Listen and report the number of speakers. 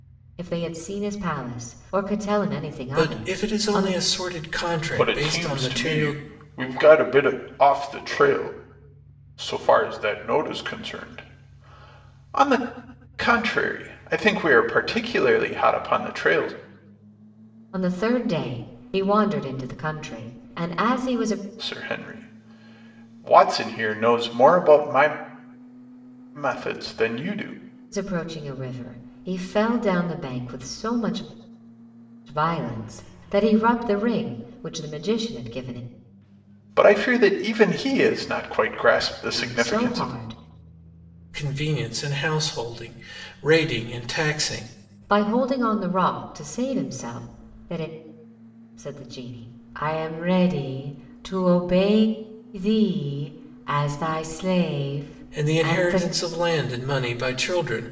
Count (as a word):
three